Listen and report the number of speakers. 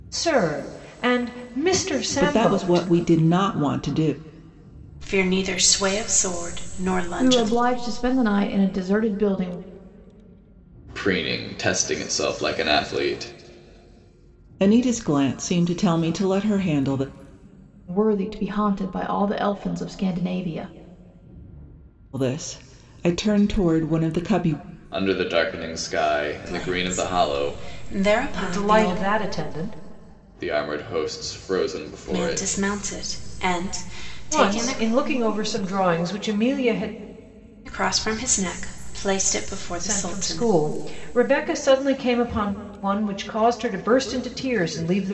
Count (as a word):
five